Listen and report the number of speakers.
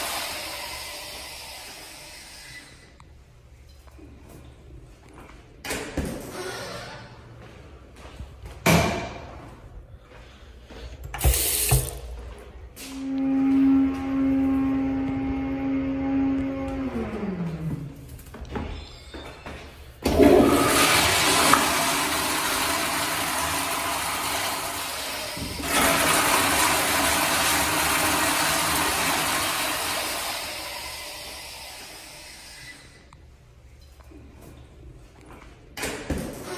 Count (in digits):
0